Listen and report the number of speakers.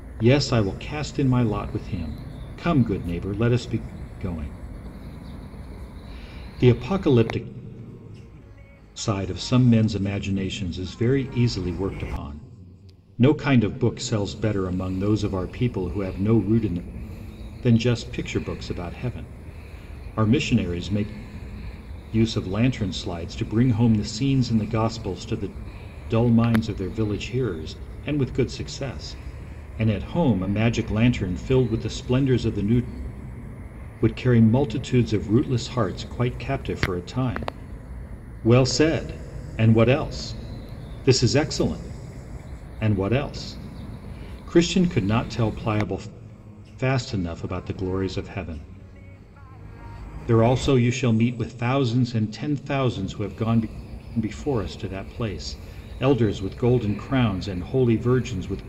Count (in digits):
1